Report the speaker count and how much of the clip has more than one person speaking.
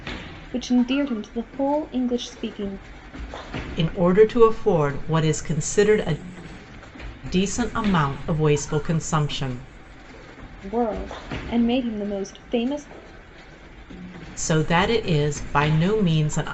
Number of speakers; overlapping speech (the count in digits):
2, no overlap